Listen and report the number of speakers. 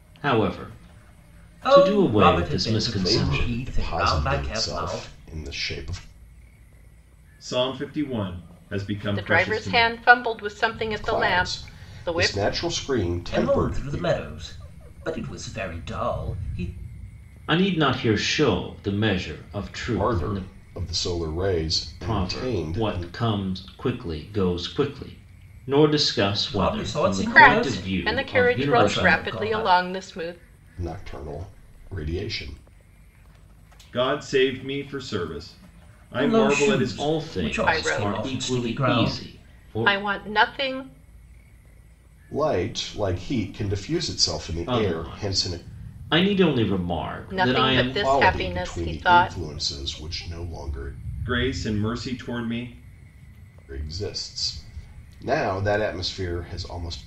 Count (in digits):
5